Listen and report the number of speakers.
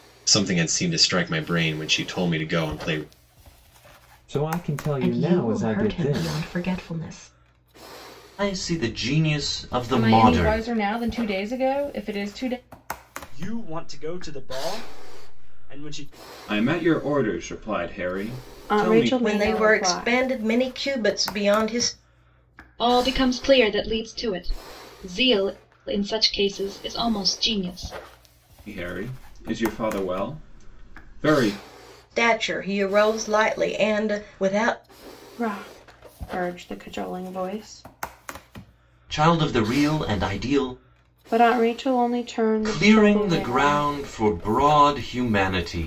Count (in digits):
10